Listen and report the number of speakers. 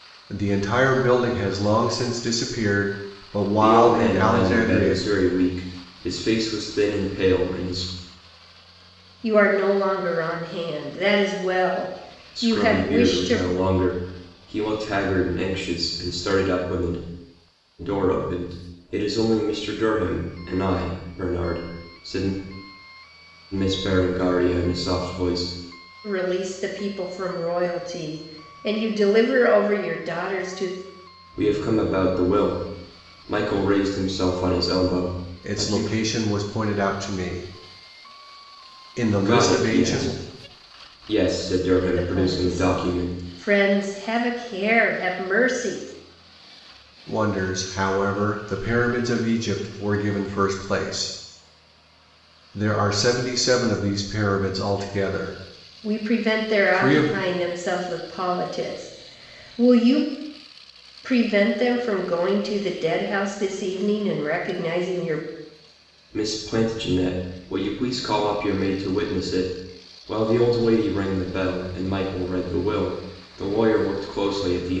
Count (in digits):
3